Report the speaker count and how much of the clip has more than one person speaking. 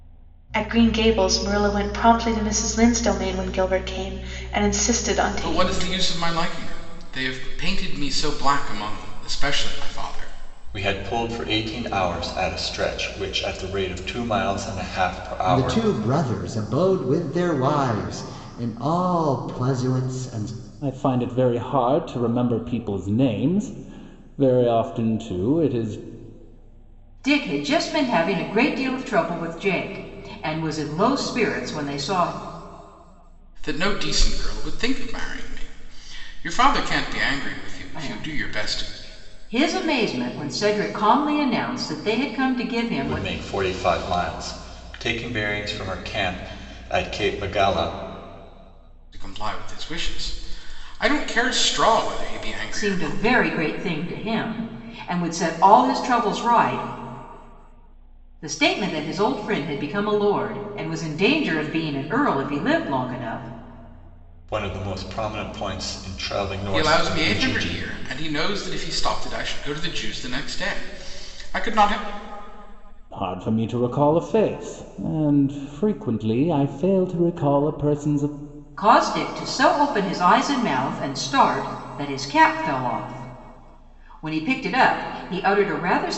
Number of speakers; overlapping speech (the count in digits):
6, about 5%